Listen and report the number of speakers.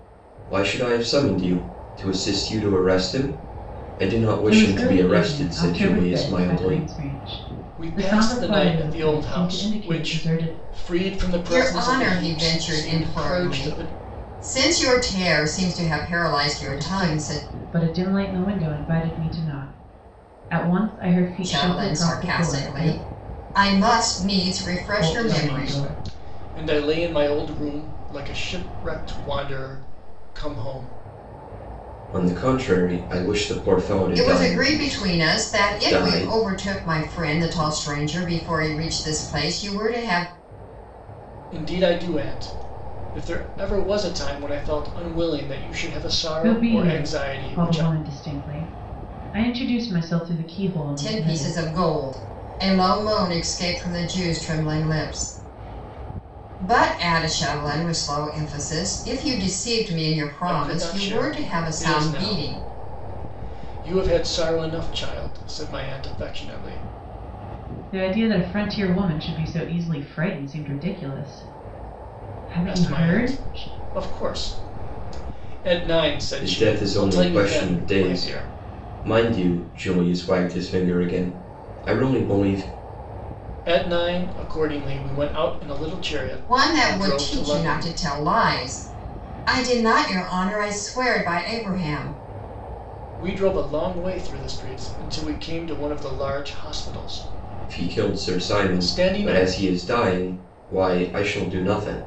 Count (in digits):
4